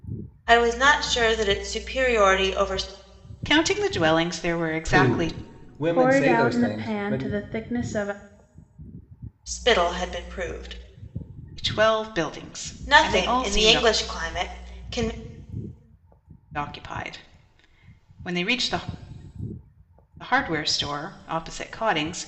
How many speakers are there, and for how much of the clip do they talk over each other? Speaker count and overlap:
4, about 14%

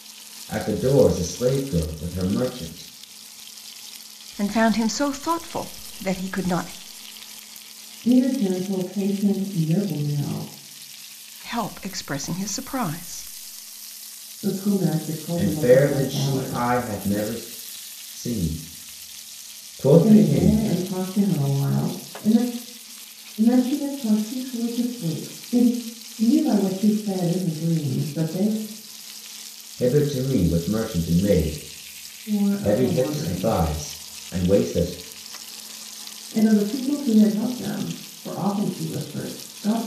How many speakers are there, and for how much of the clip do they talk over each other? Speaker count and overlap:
3, about 8%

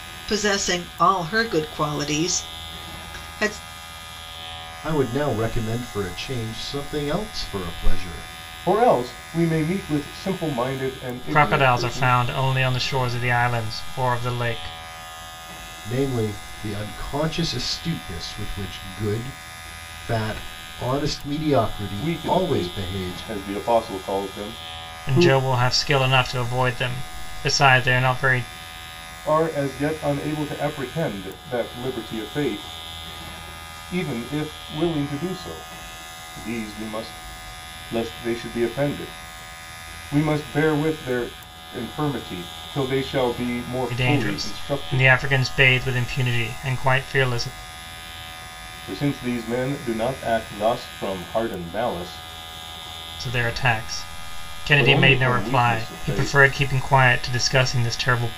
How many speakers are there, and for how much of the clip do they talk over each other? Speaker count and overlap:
4, about 9%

